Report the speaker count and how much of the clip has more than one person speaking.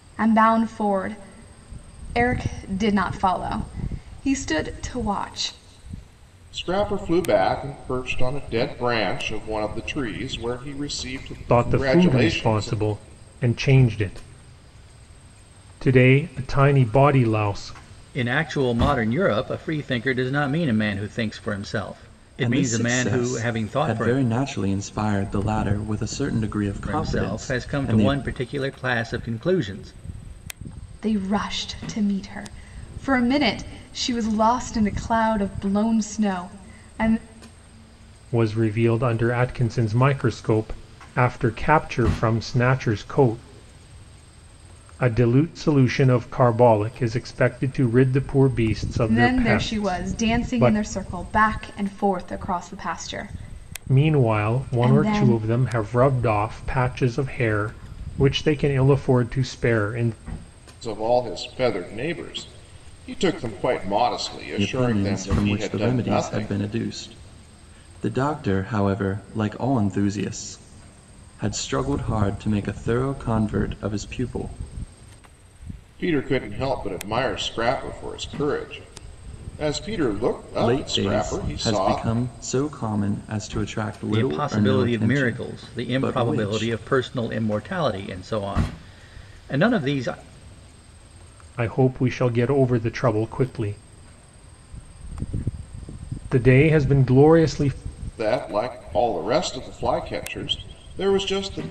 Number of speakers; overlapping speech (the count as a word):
five, about 14%